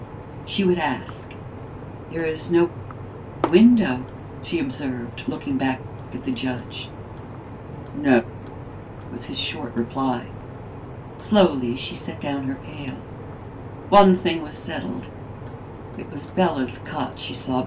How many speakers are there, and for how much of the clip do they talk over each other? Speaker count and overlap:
1, no overlap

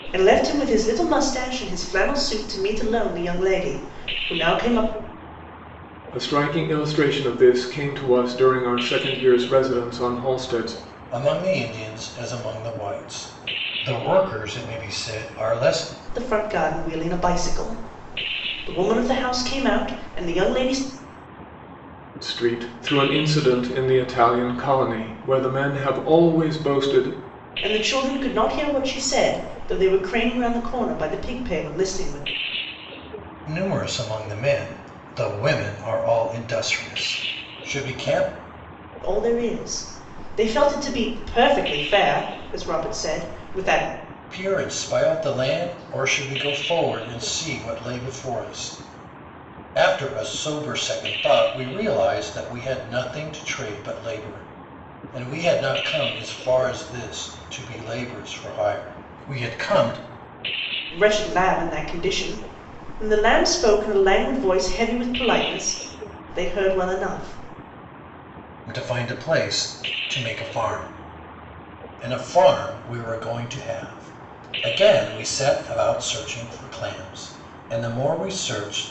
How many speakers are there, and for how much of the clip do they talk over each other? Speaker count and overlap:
3, no overlap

